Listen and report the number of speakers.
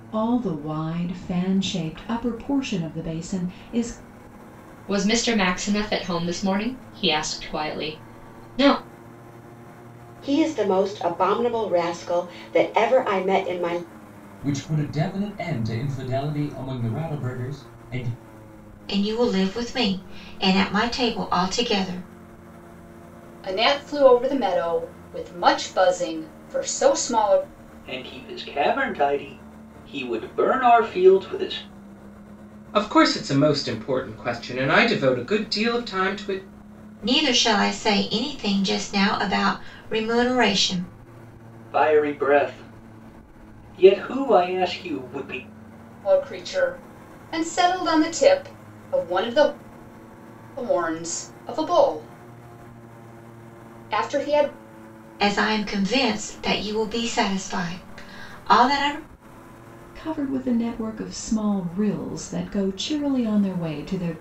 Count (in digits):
8